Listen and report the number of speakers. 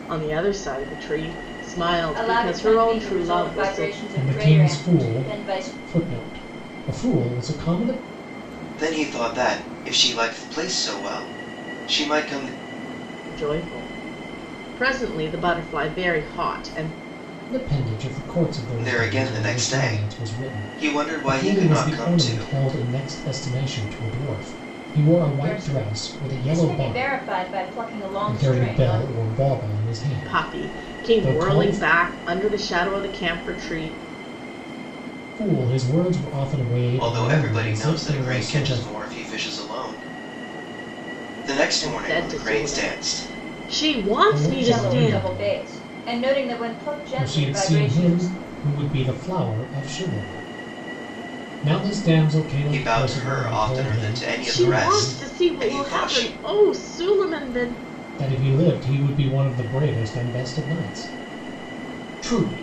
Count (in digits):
4